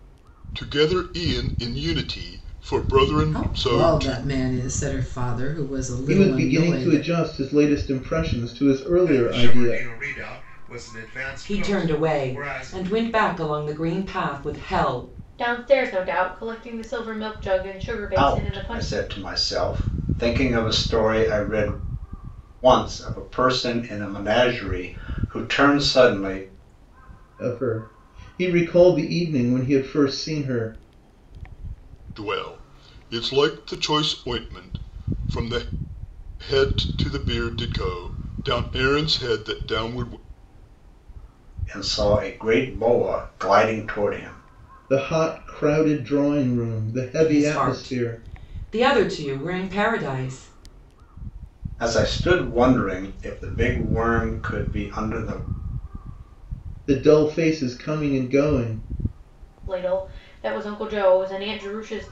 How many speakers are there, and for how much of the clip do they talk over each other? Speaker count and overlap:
7, about 10%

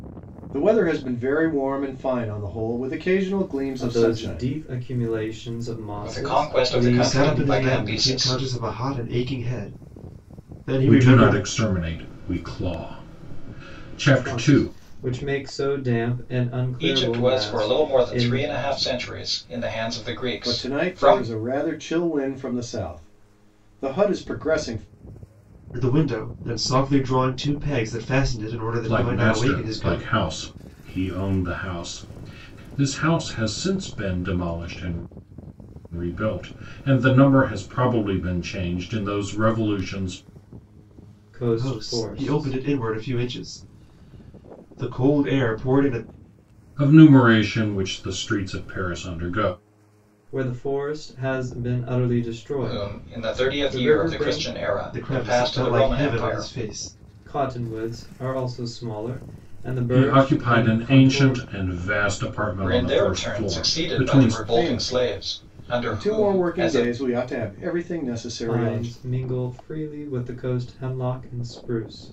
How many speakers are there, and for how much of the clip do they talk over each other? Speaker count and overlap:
5, about 27%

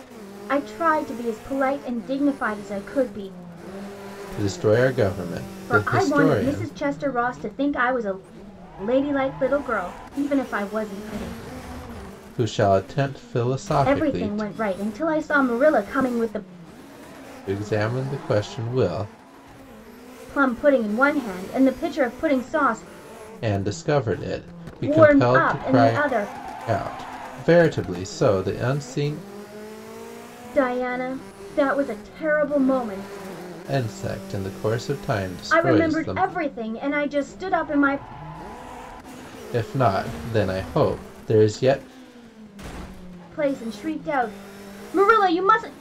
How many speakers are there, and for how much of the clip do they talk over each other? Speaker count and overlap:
2, about 8%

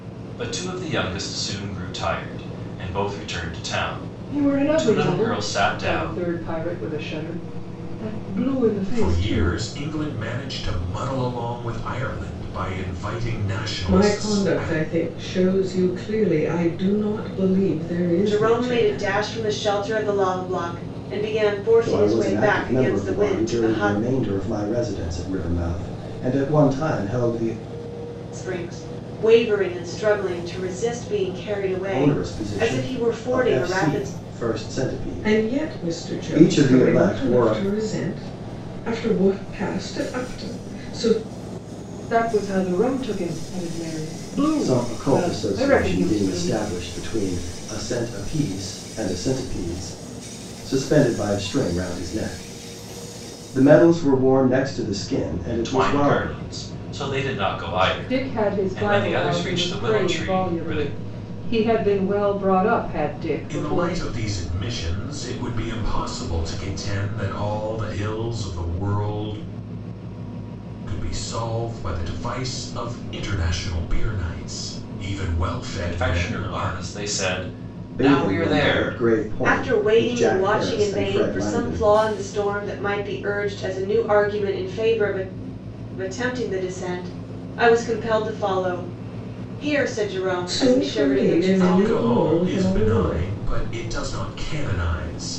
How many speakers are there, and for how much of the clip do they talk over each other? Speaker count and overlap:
6, about 26%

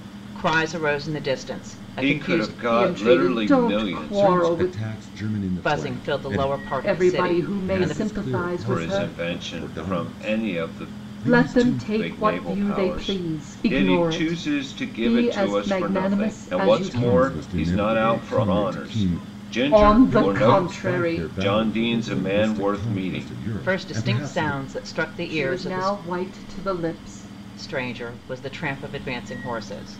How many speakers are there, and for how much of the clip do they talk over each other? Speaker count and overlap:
4, about 71%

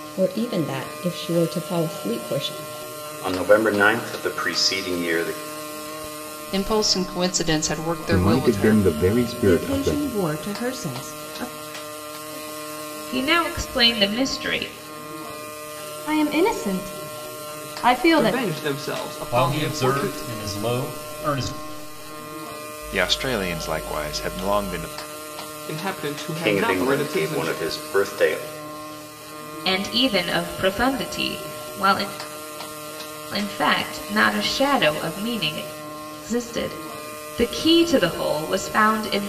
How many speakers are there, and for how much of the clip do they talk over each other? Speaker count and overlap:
10, about 11%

